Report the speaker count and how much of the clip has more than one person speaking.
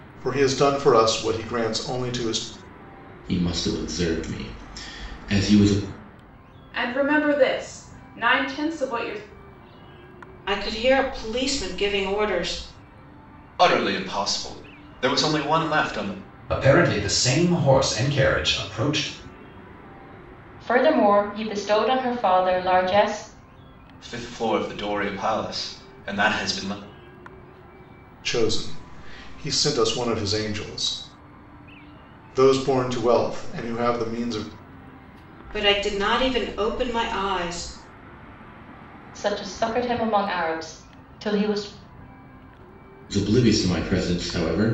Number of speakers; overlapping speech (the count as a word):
seven, no overlap